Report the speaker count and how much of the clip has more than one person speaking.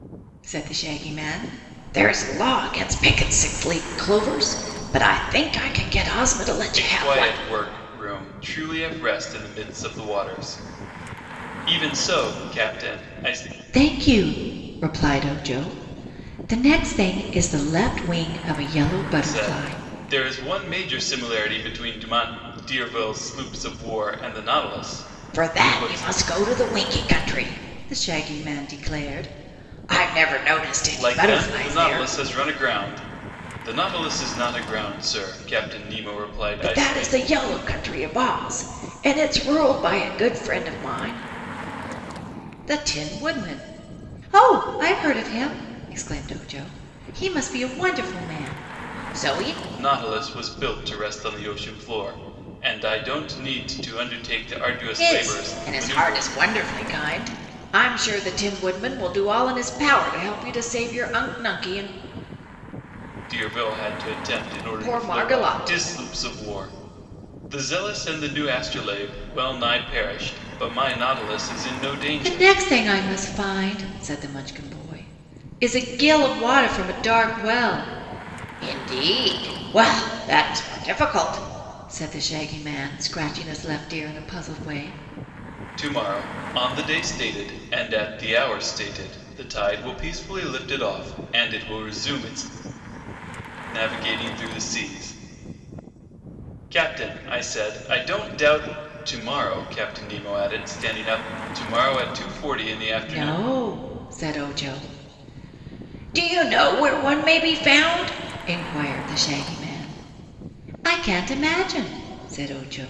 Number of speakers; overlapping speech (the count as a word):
two, about 7%